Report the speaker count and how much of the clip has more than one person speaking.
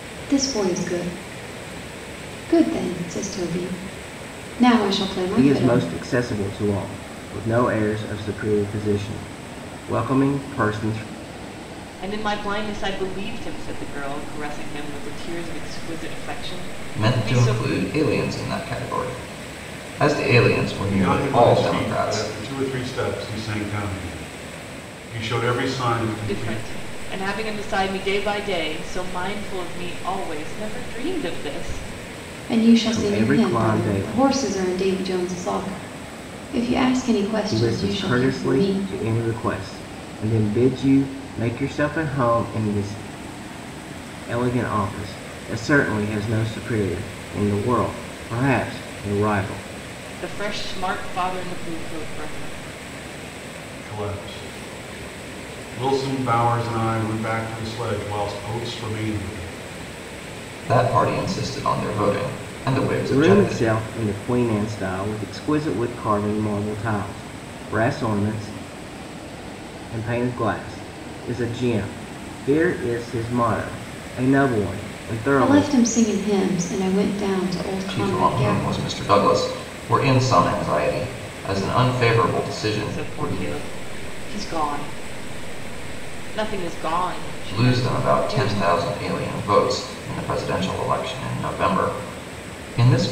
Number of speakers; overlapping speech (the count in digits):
5, about 11%